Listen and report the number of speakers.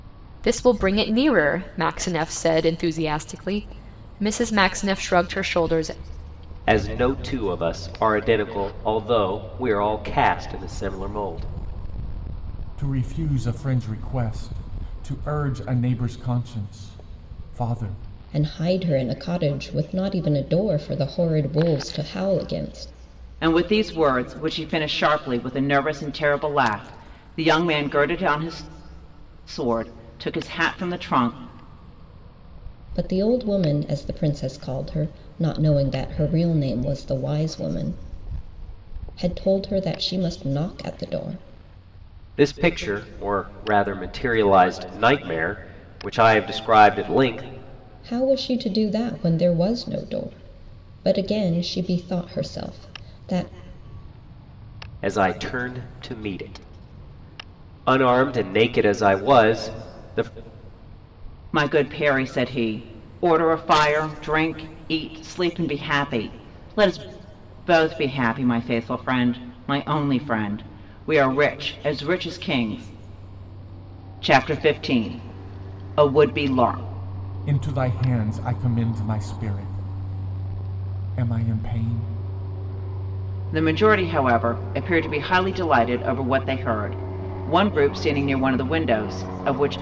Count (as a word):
five